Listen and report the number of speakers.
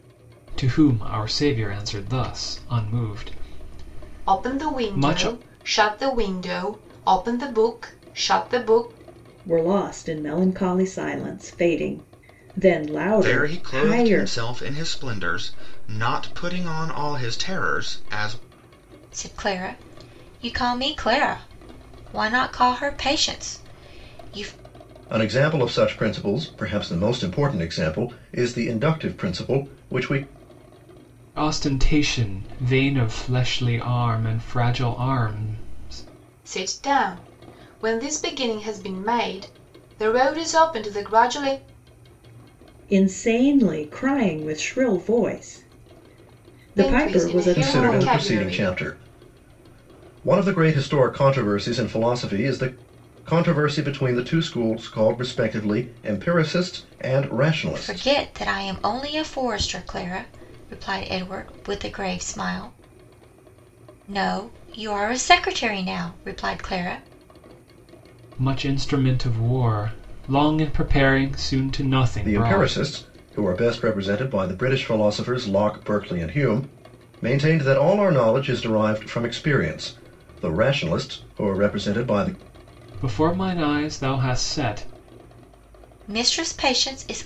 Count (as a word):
six